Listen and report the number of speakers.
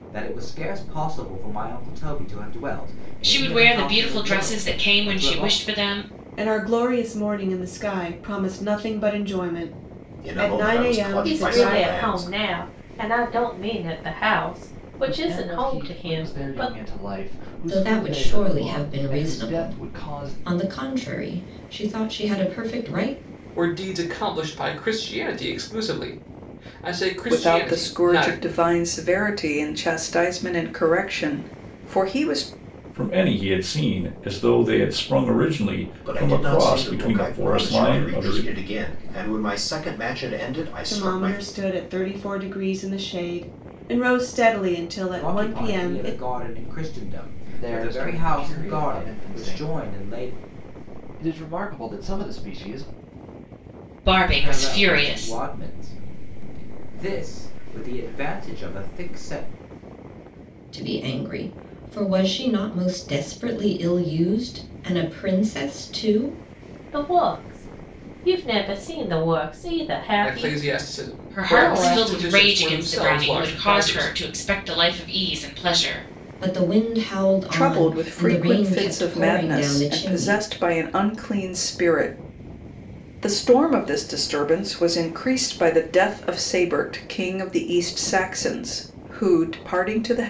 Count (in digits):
10